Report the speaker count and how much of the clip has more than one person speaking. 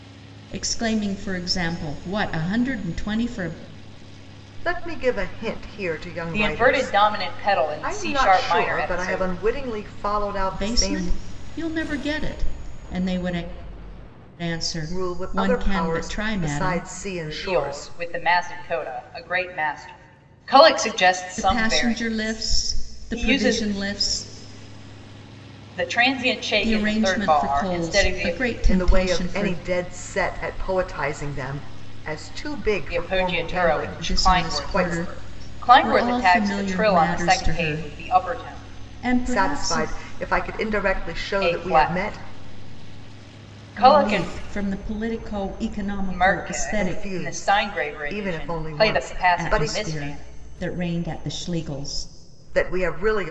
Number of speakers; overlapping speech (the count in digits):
3, about 43%